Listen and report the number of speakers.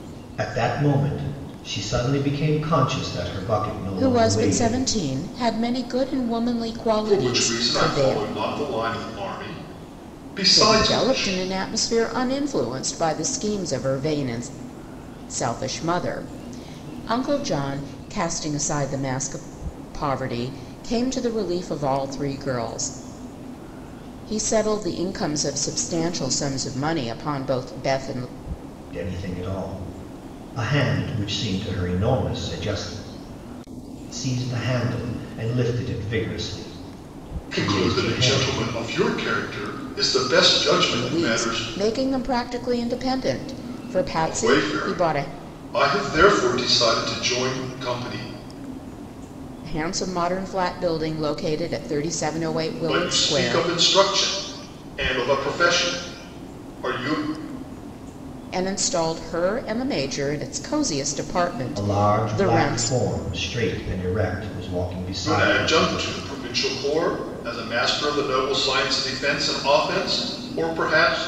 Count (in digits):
3